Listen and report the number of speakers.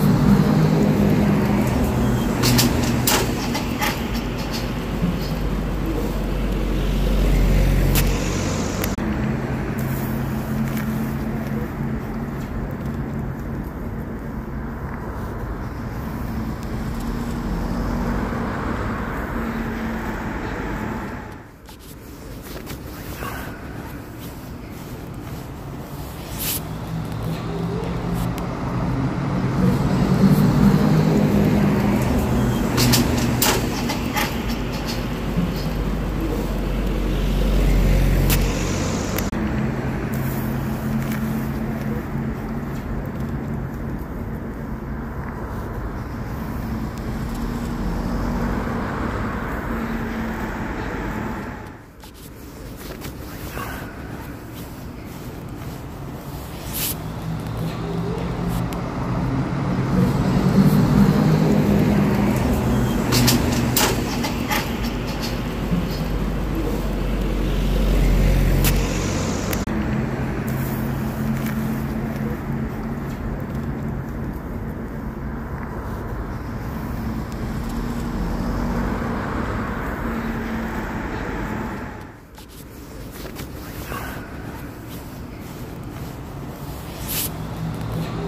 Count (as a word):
zero